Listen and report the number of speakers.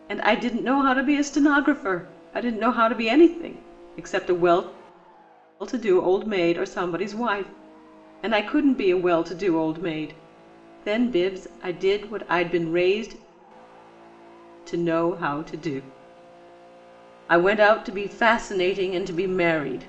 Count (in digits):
1